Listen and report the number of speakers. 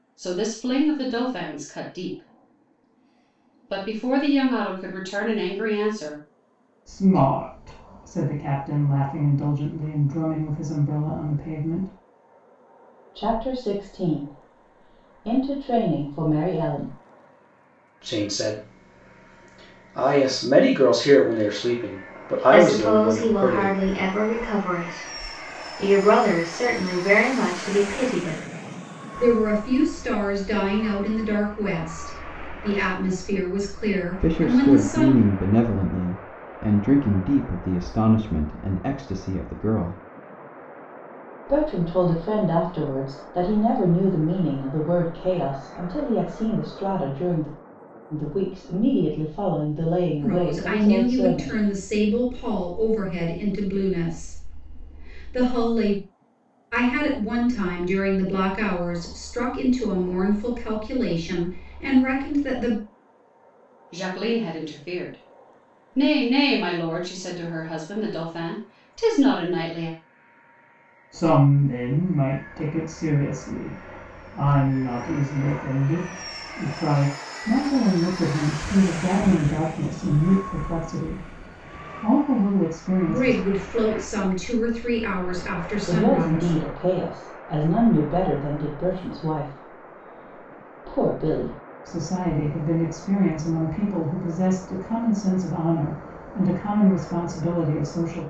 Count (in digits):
7